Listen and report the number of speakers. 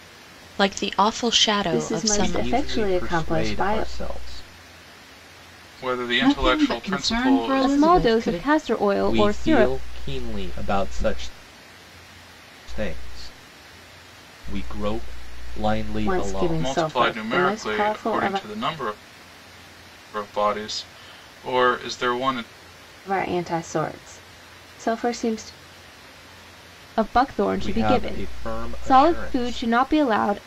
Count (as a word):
six